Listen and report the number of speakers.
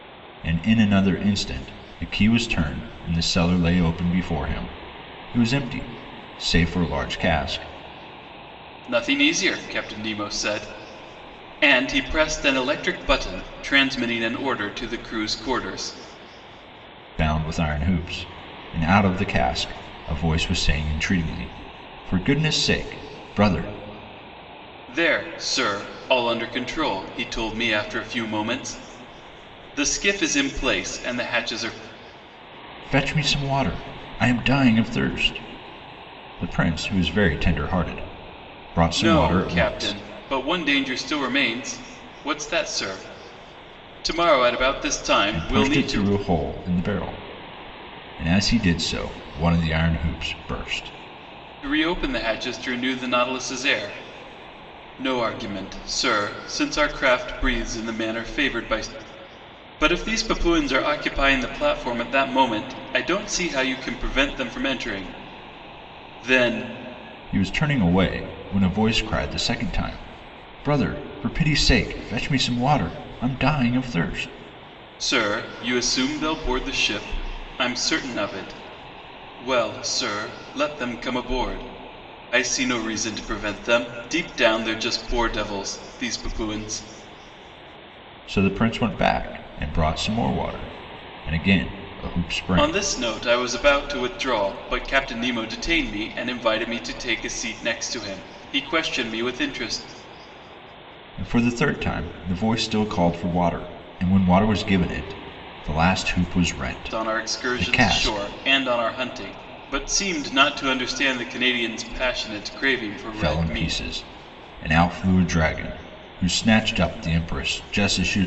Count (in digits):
2